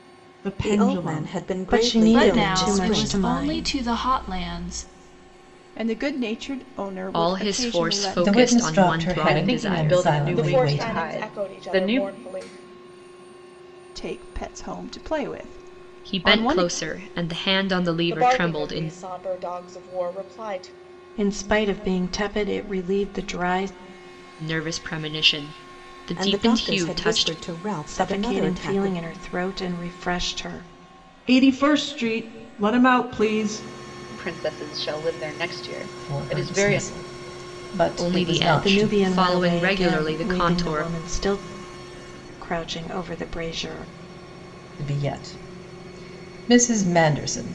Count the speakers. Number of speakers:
9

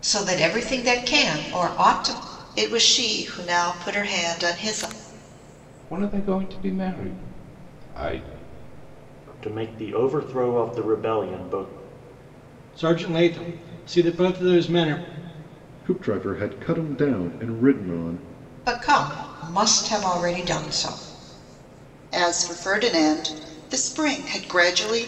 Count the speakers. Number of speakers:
6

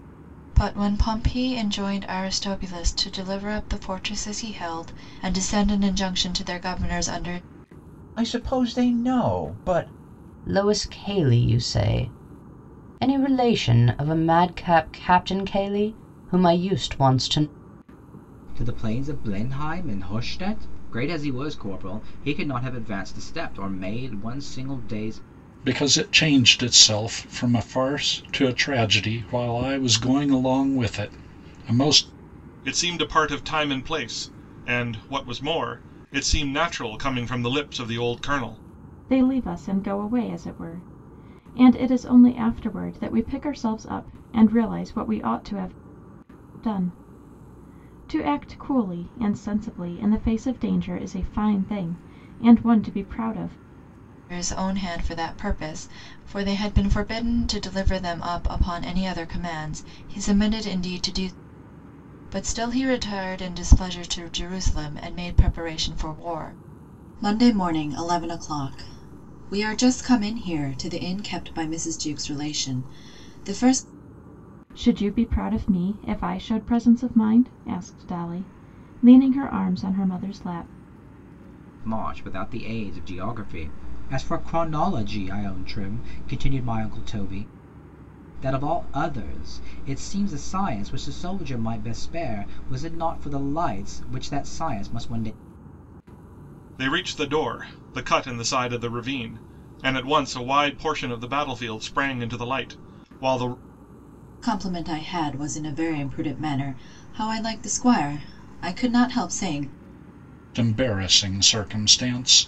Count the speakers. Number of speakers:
7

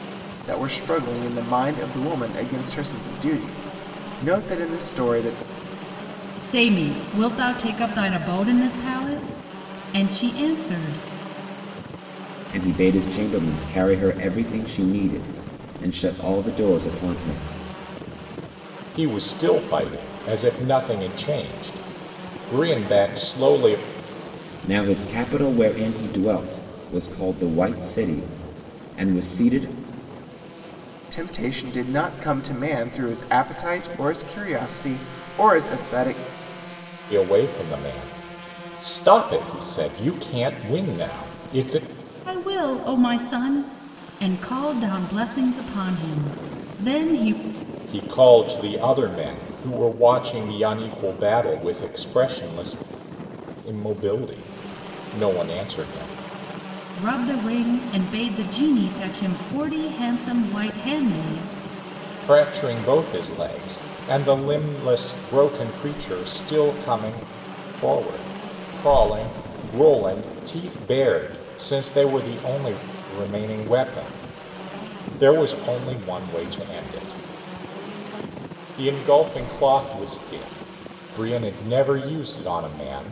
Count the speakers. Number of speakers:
4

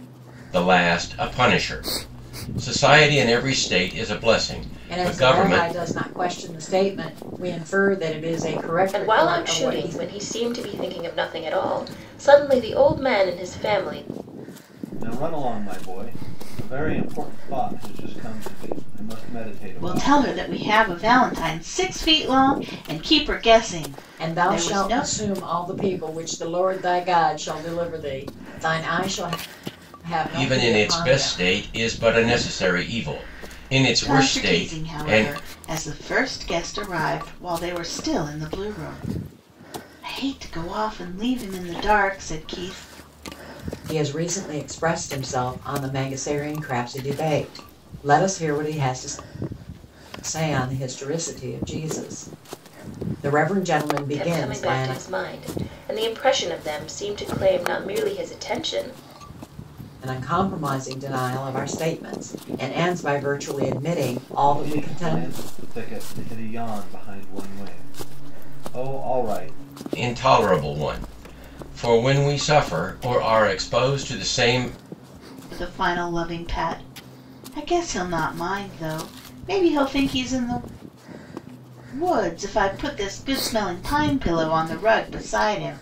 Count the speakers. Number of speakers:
5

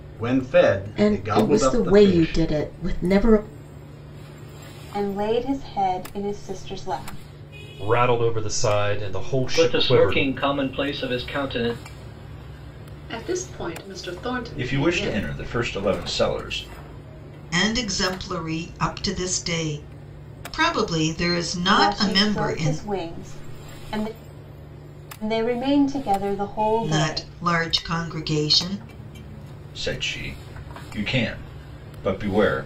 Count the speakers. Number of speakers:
8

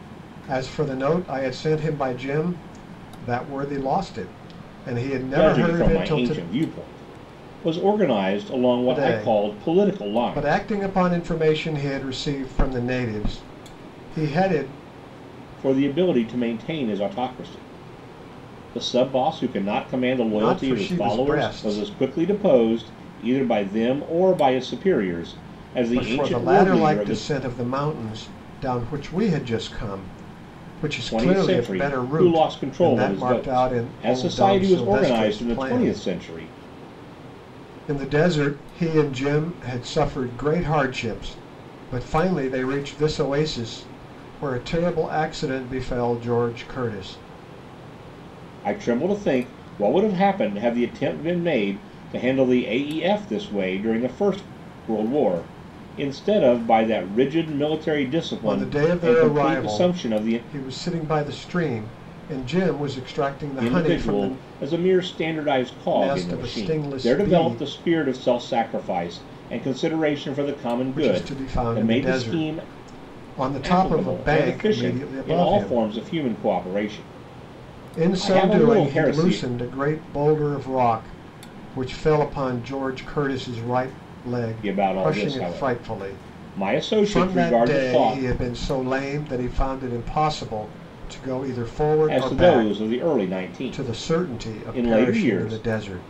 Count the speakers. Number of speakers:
2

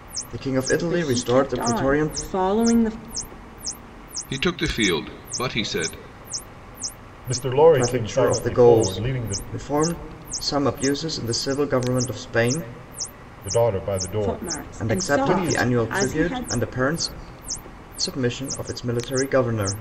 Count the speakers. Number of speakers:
4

